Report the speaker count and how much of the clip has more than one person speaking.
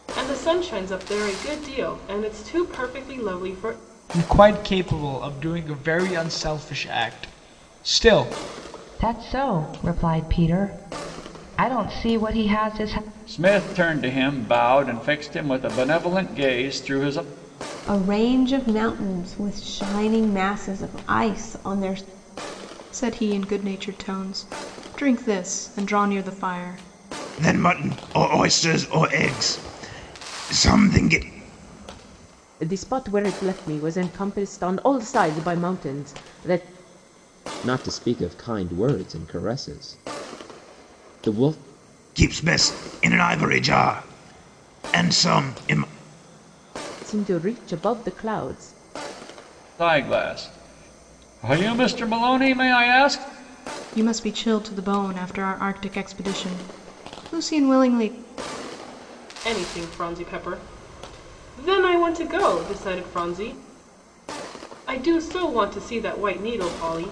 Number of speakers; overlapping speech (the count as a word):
nine, no overlap